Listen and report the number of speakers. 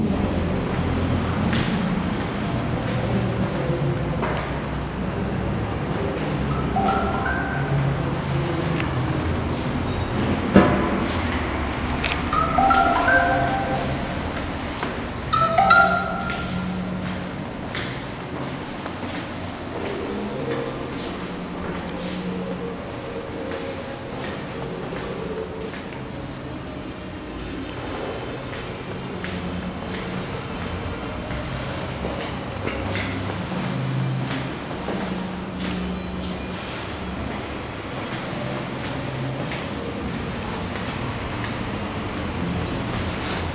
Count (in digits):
0